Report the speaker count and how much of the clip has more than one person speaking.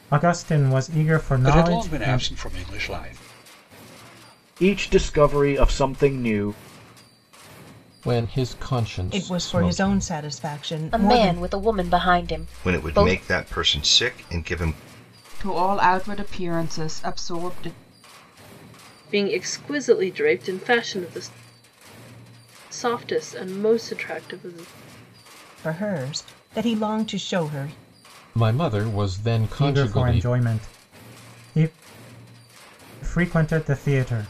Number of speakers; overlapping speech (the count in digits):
9, about 11%